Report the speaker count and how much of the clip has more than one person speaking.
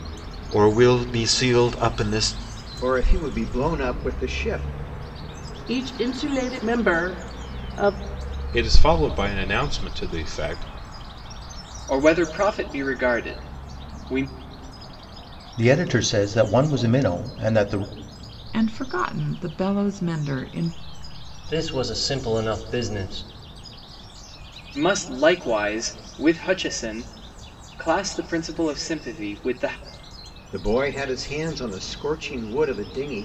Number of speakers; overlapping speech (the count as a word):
eight, no overlap